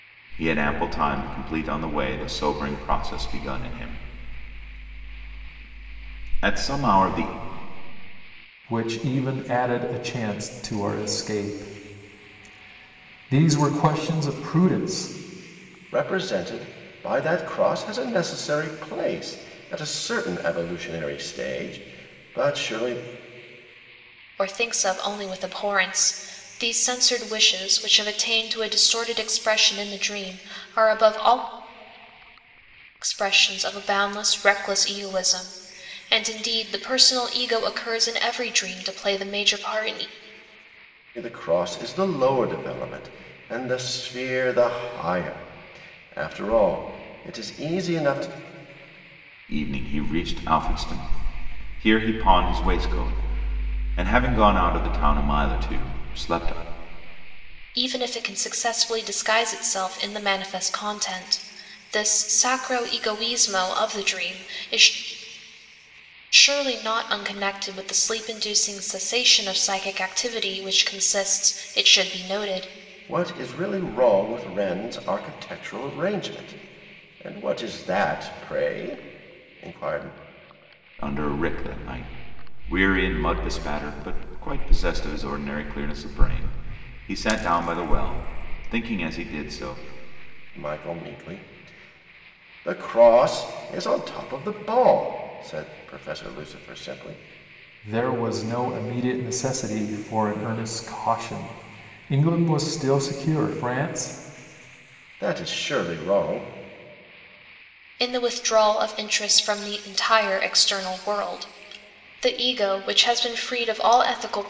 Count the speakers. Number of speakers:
4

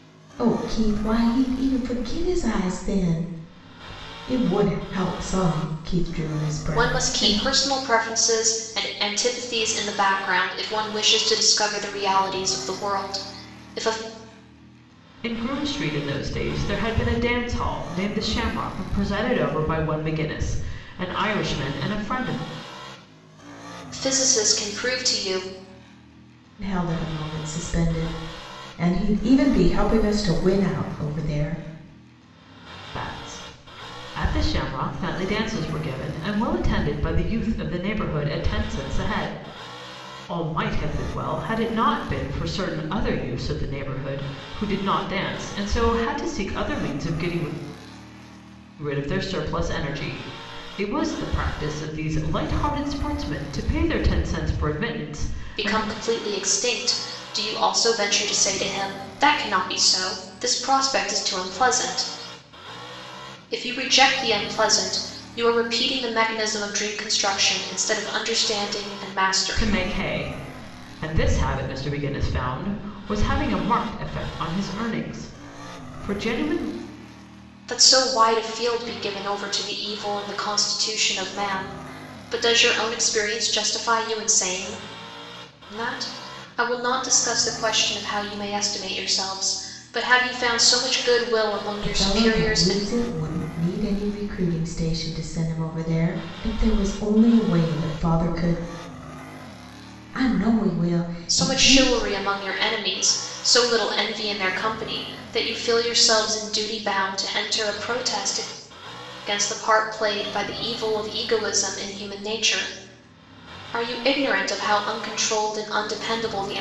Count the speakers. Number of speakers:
3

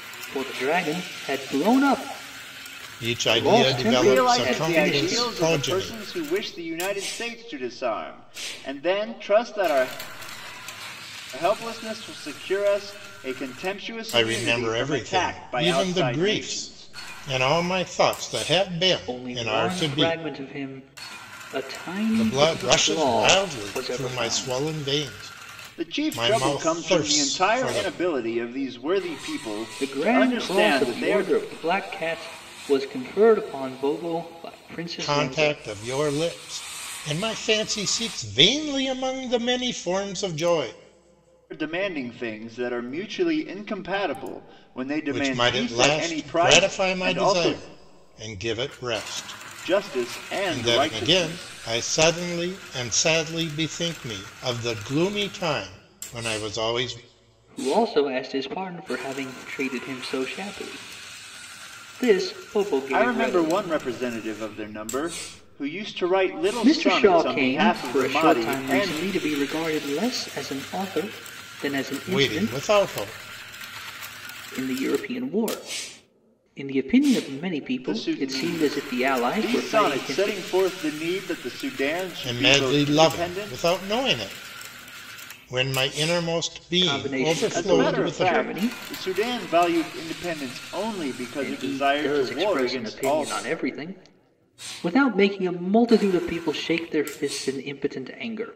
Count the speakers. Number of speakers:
3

